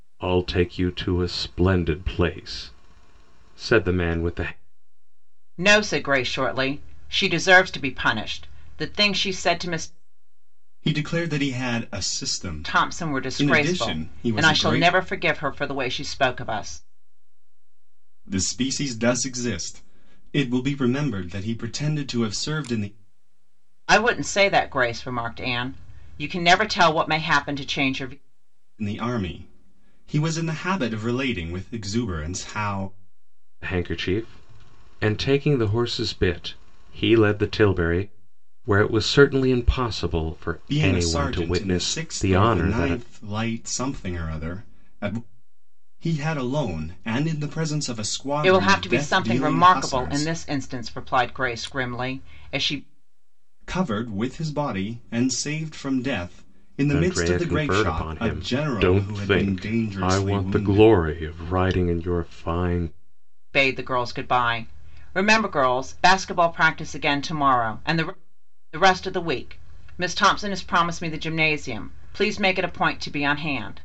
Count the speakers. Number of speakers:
3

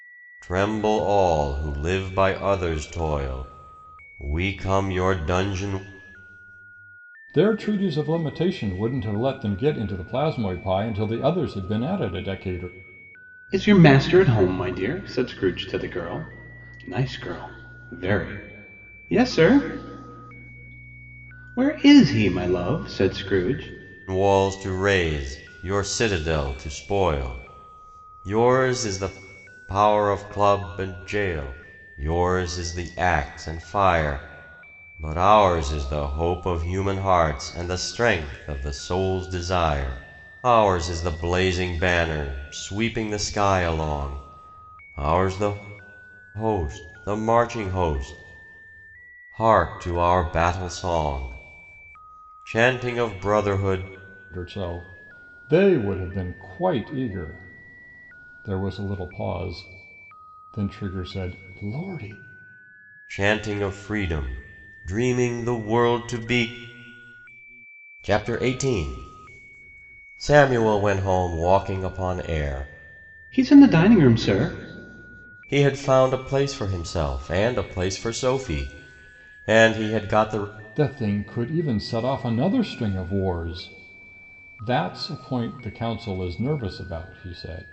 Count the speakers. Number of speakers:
3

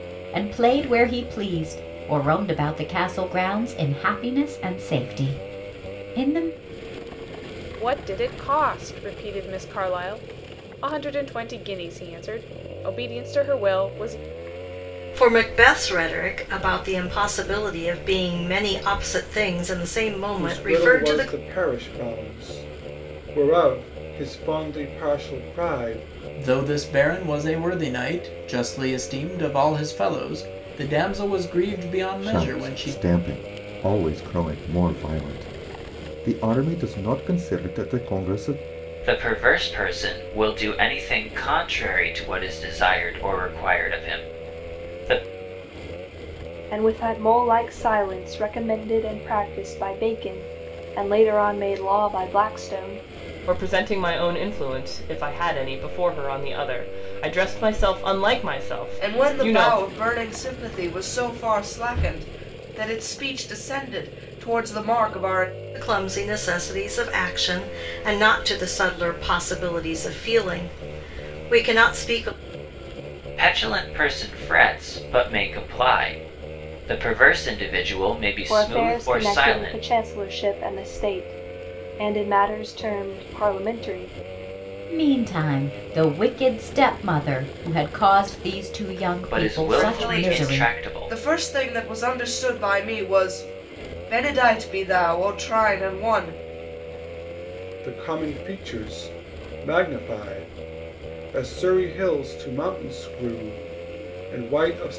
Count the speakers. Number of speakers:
10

